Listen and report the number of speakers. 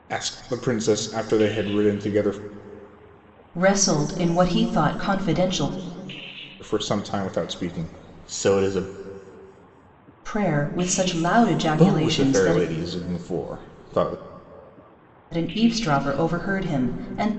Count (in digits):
2